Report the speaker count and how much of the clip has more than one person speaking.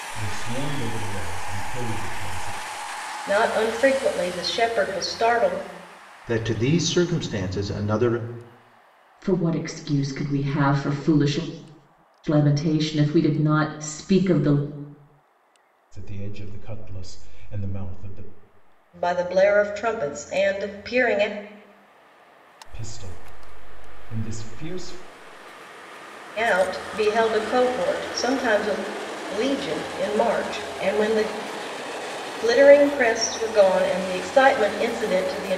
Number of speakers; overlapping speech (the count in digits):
4, no overlap